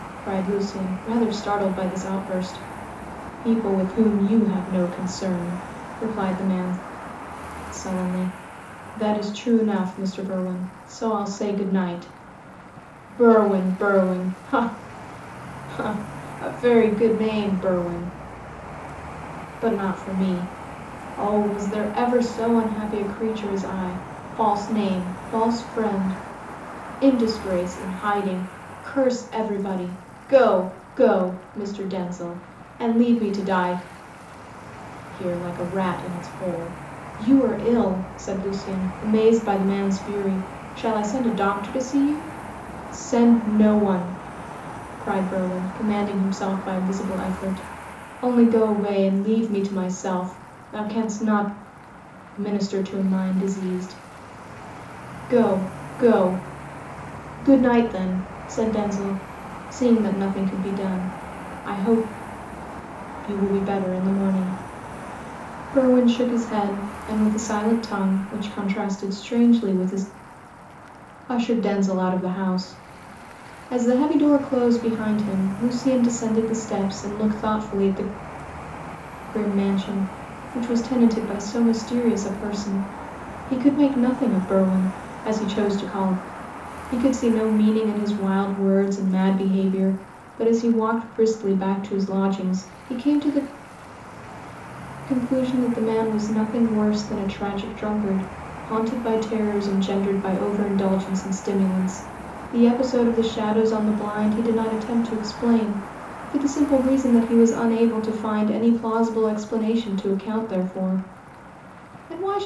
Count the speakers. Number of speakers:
one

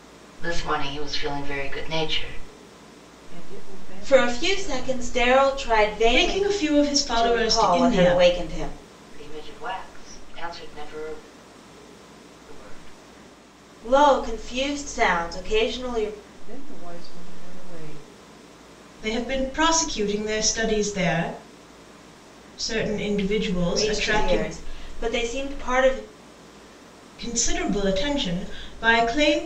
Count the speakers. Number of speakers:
four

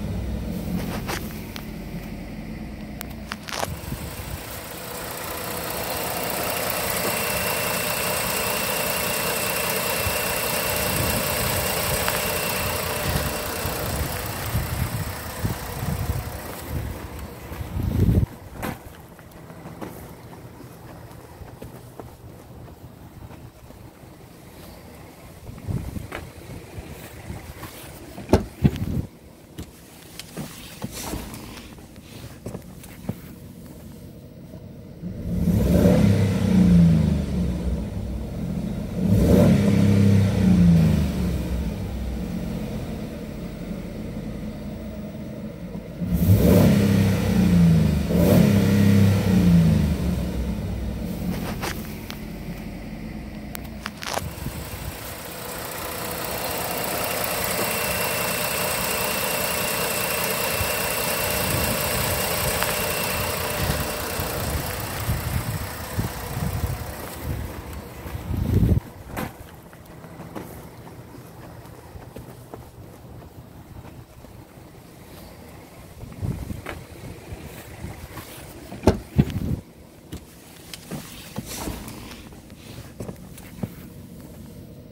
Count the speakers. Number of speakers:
zero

